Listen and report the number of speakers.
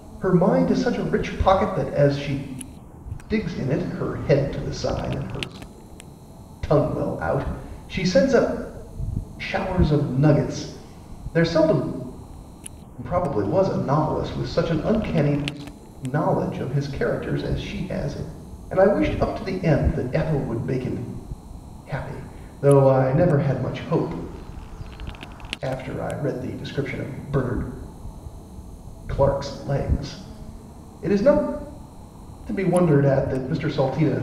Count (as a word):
one